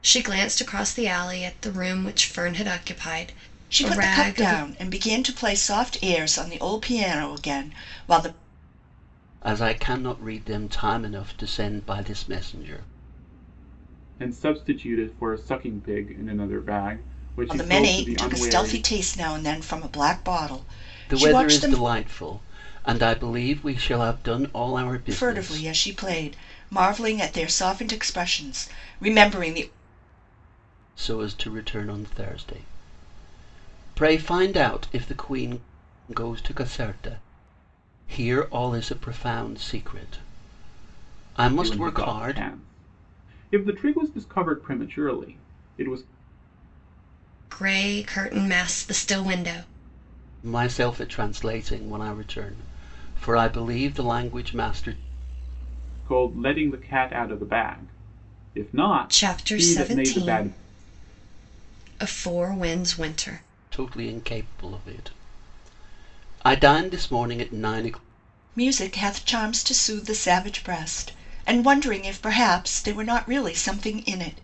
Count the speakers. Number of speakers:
4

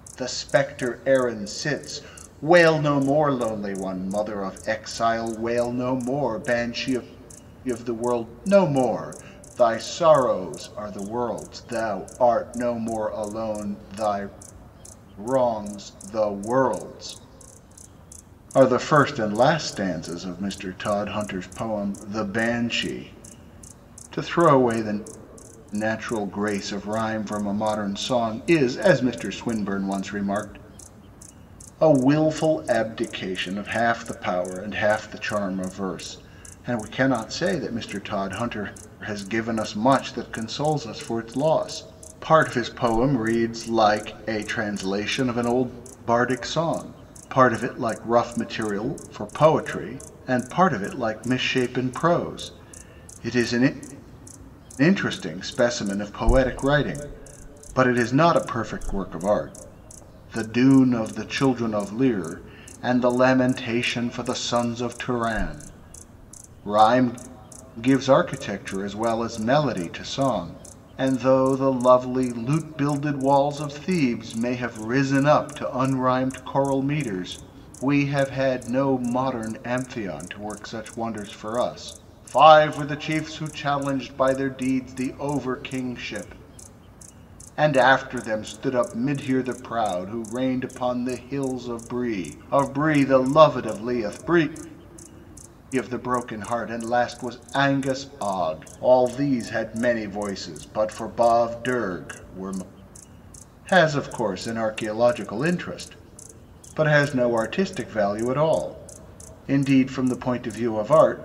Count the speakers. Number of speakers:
1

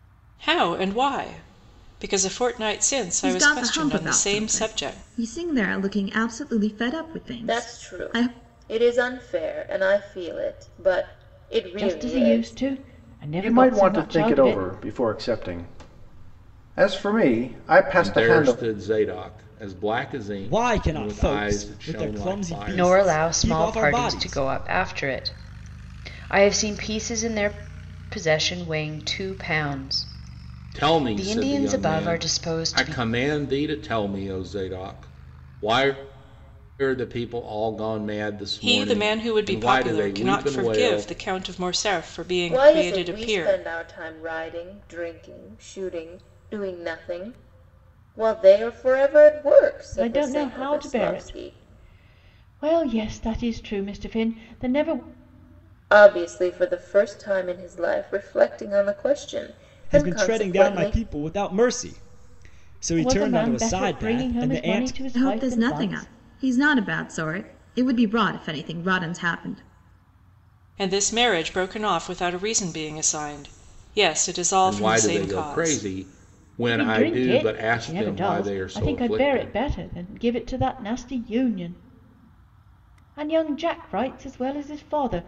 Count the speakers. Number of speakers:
8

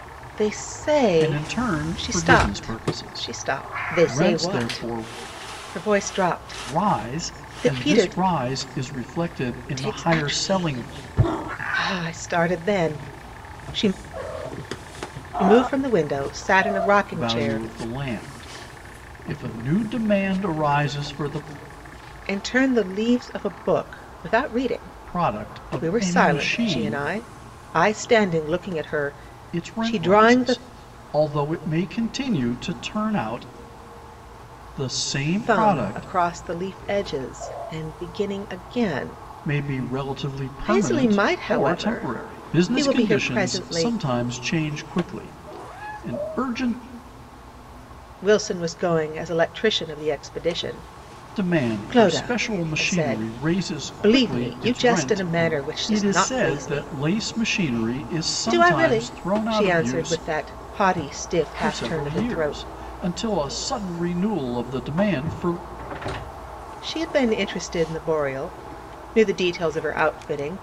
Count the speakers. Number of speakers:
2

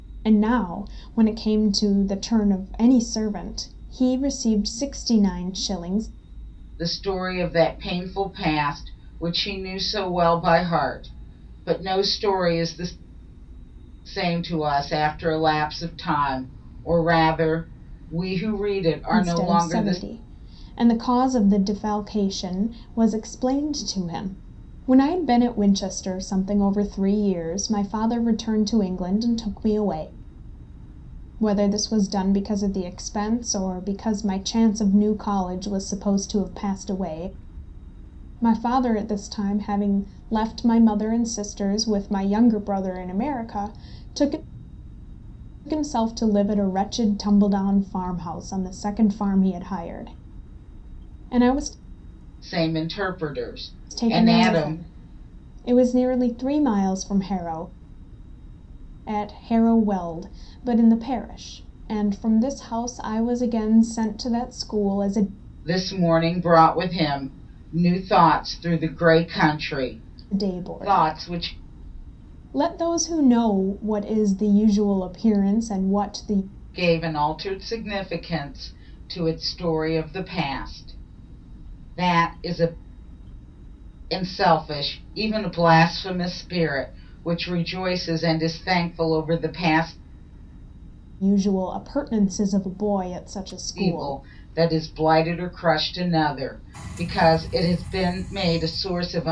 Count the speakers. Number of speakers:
2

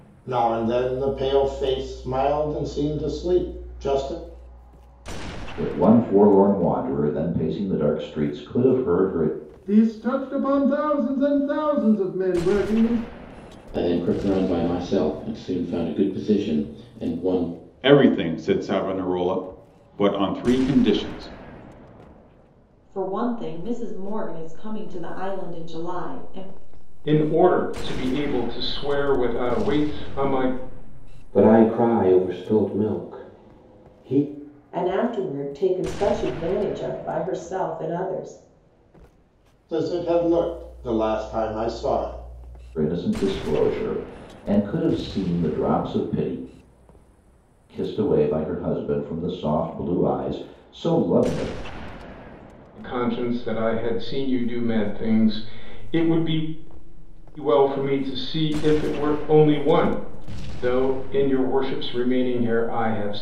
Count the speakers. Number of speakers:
9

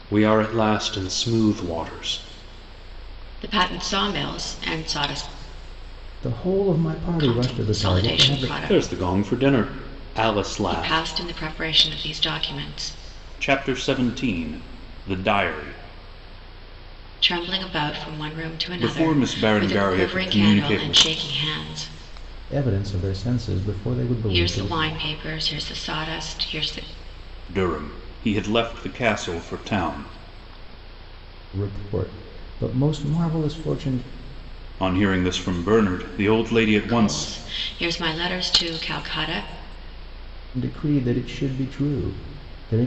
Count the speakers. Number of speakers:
3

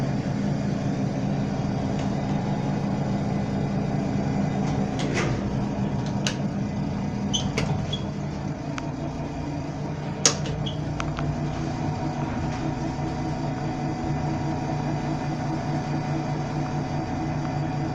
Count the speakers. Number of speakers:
0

